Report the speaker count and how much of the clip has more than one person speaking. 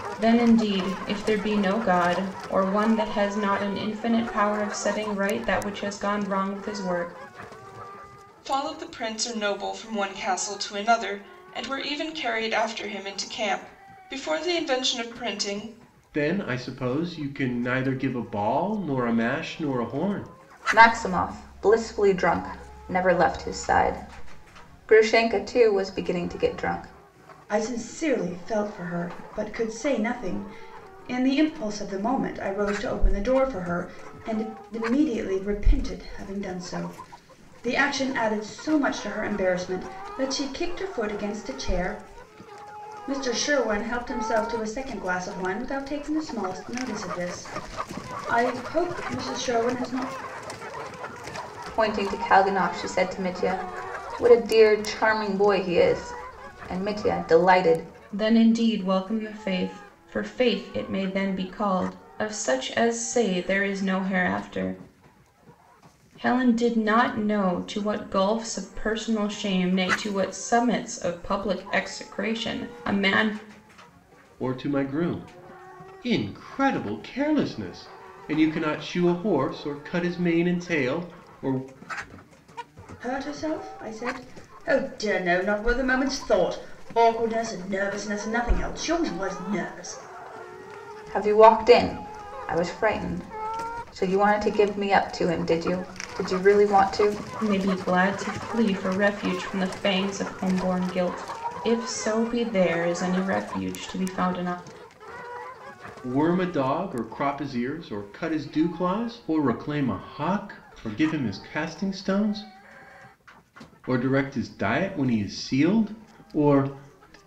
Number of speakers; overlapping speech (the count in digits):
5, no overlap